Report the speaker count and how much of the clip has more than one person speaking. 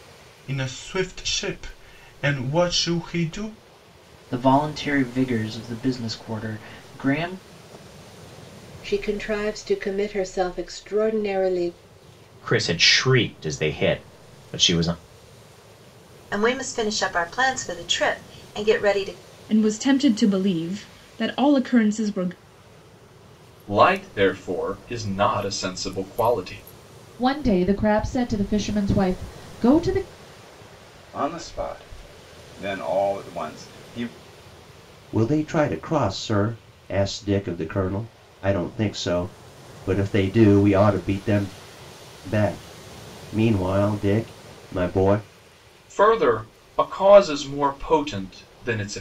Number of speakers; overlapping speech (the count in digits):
10, no overlap